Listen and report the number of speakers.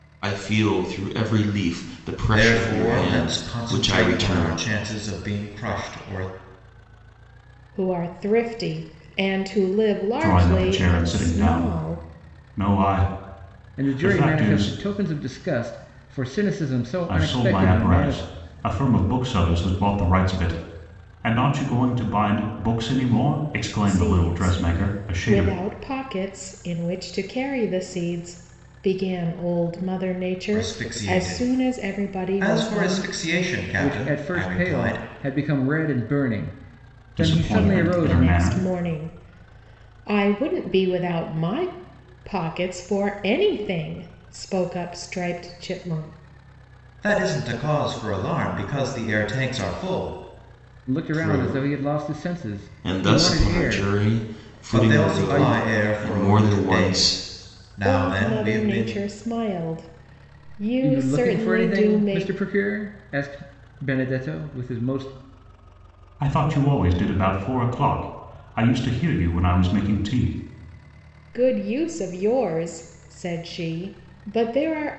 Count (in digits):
5